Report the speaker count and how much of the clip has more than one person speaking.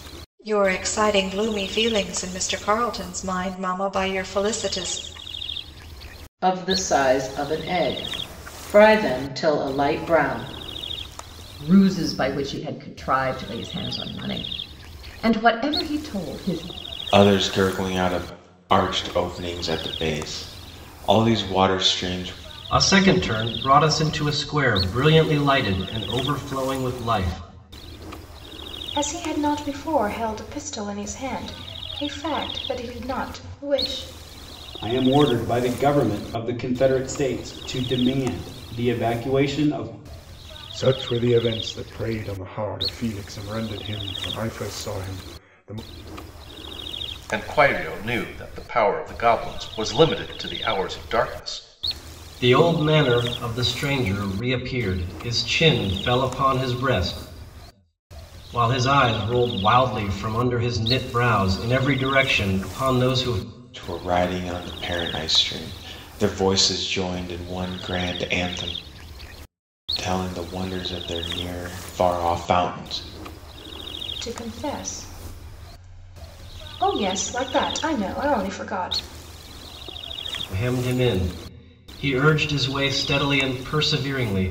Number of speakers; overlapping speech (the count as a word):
nine, no overlap